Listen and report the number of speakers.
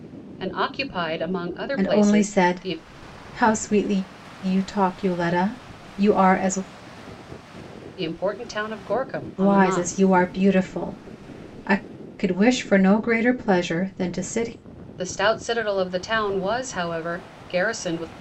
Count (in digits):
2